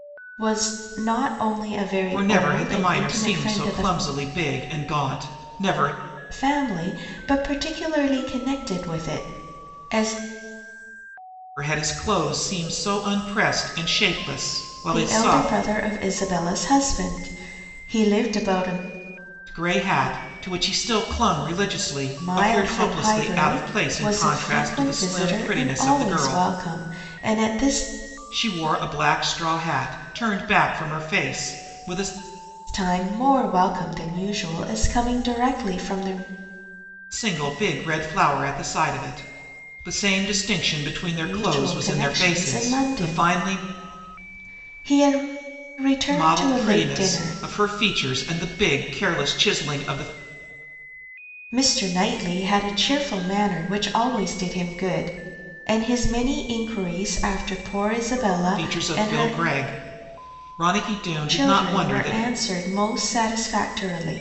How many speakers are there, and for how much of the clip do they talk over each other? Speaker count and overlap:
2, about 19%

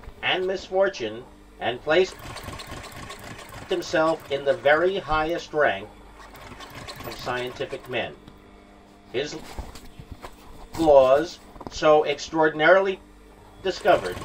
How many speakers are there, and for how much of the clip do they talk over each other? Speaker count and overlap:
1, no overlap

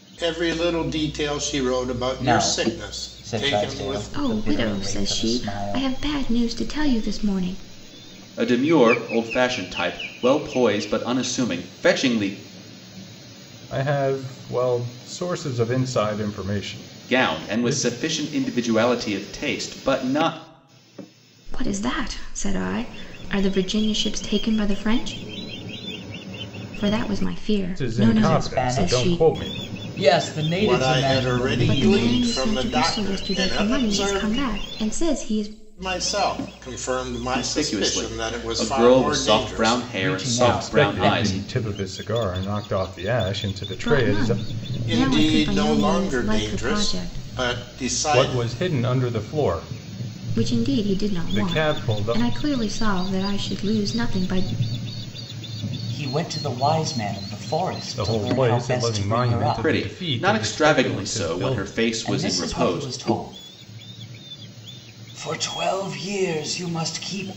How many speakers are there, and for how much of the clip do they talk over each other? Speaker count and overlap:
5, about 37%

